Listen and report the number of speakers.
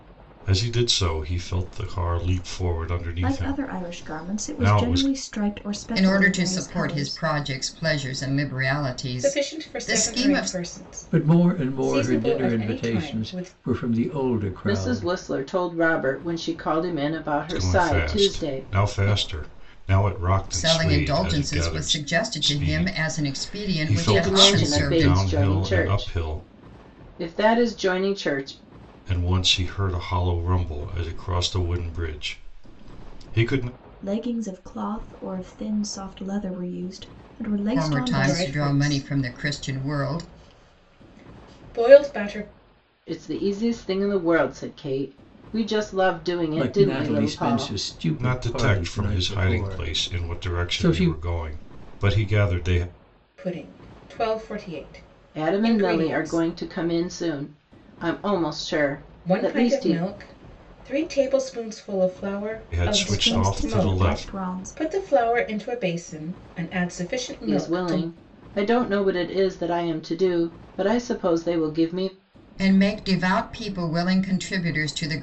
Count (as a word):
six